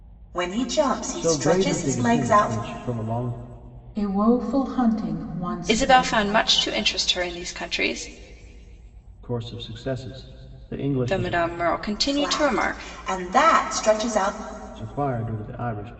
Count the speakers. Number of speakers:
4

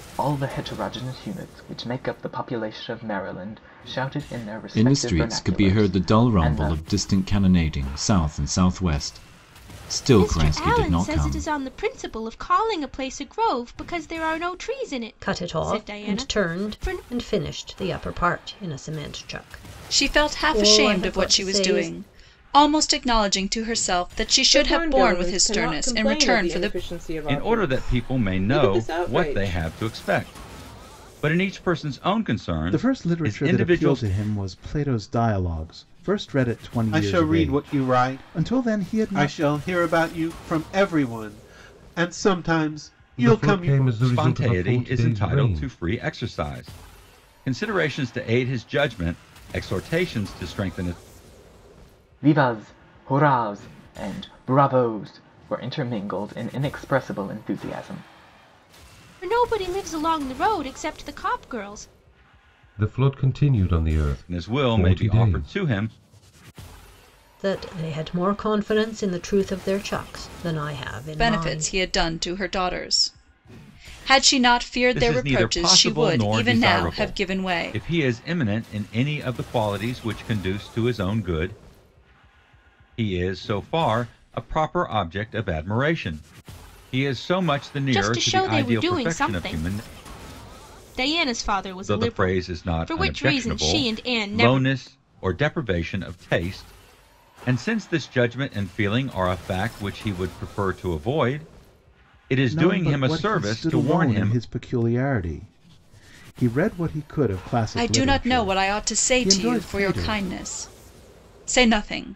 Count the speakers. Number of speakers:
10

